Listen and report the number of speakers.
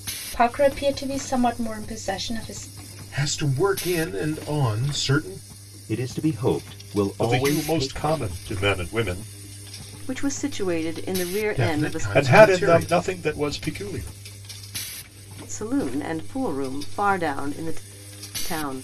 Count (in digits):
5